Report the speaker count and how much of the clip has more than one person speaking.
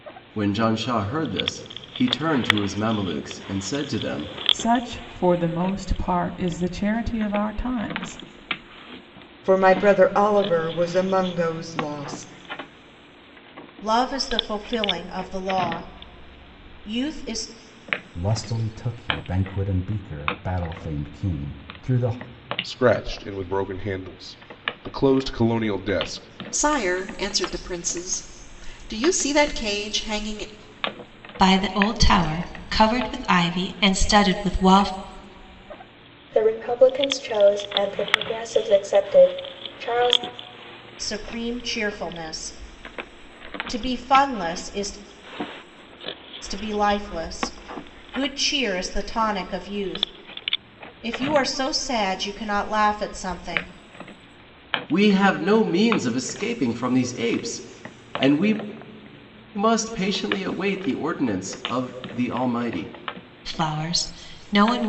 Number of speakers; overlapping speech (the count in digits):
9, no overlap